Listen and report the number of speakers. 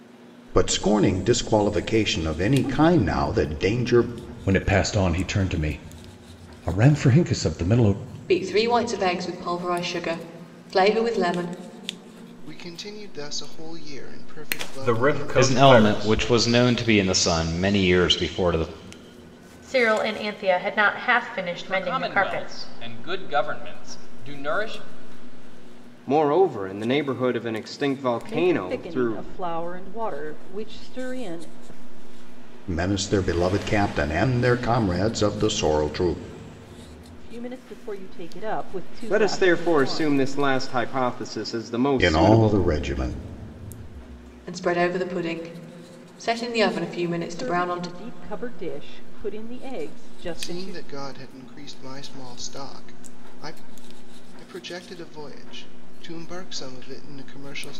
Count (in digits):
10